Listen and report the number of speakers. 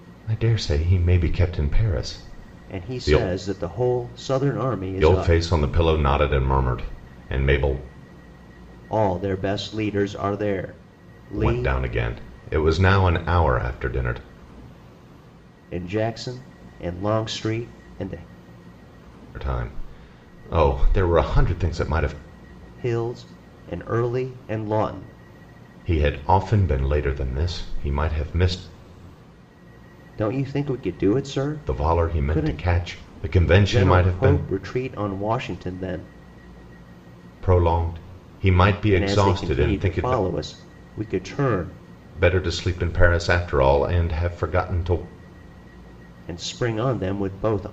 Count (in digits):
2